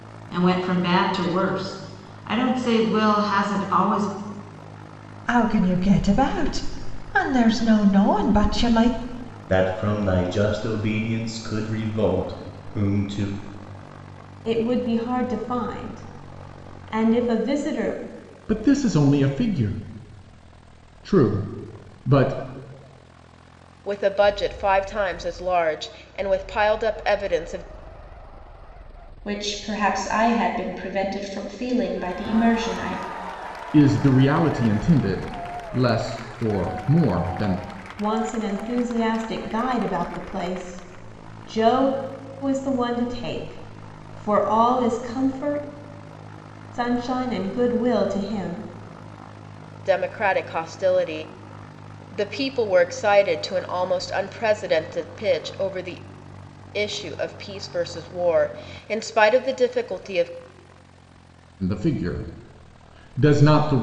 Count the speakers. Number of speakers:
7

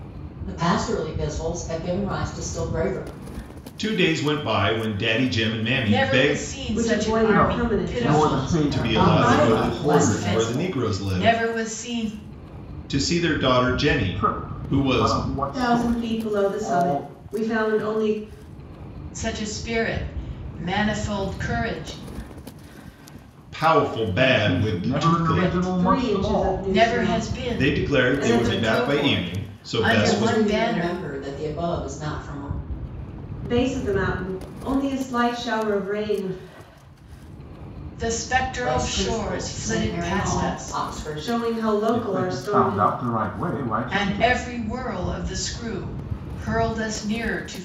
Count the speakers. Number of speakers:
5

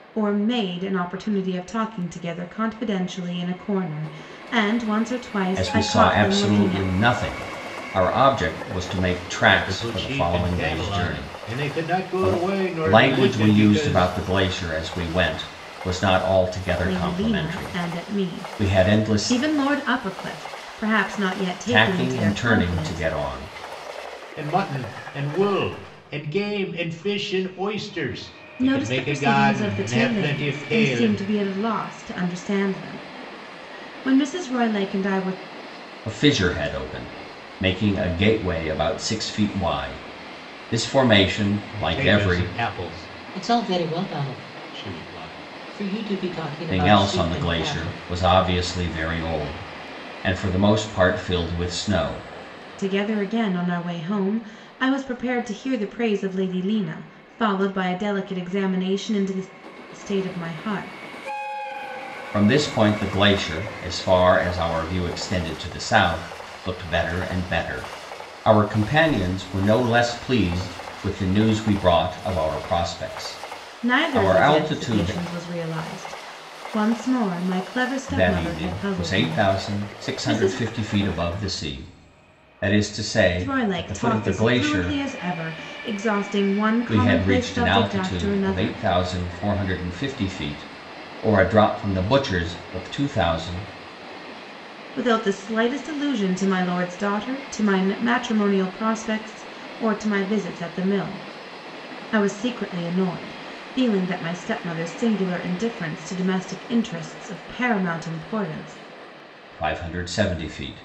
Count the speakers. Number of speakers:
3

